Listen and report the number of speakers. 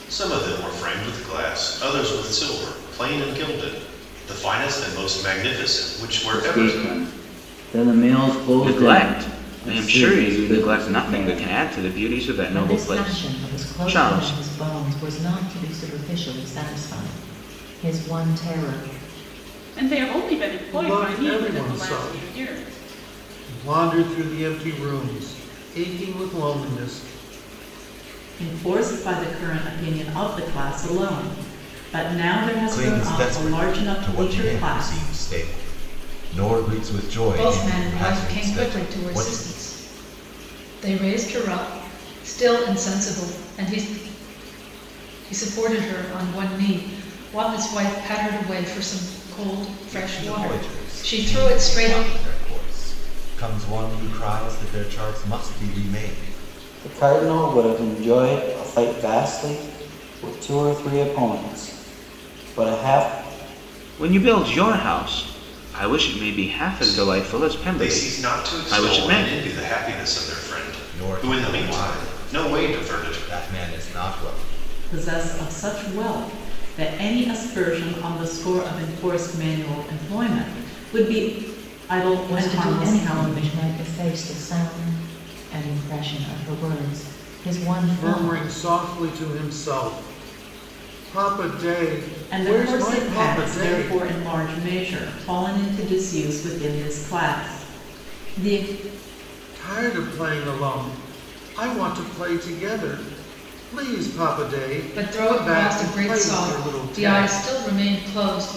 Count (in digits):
9